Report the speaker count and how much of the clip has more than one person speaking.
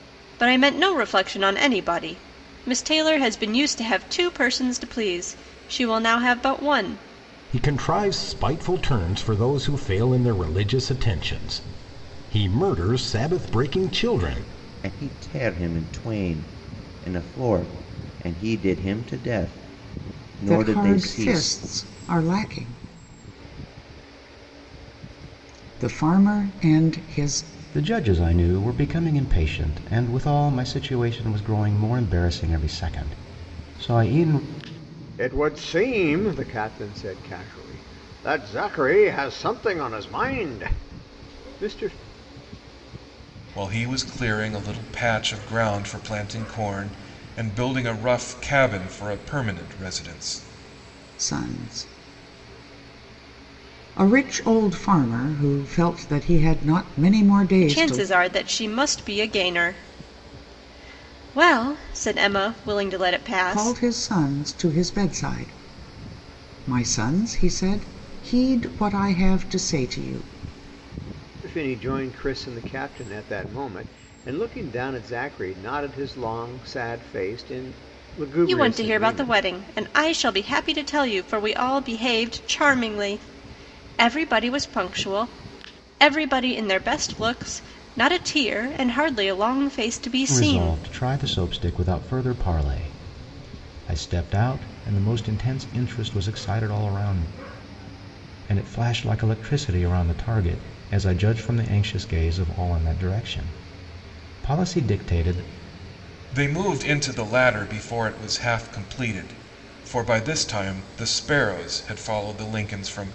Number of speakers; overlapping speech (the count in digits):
7, about 3%